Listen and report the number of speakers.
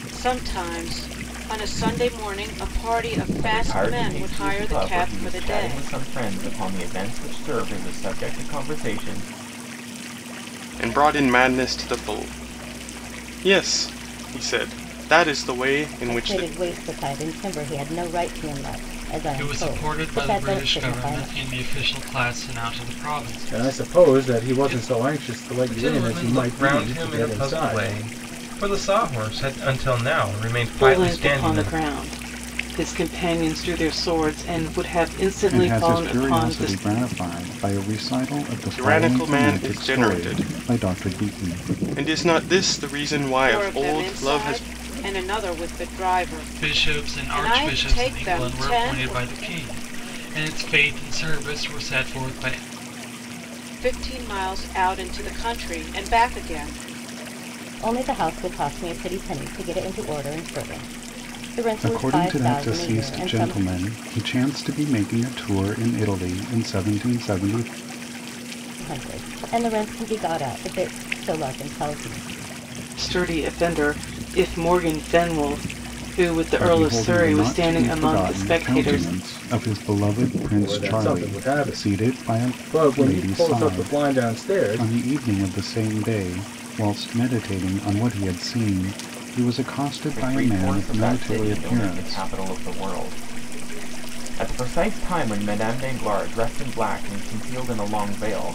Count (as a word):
nine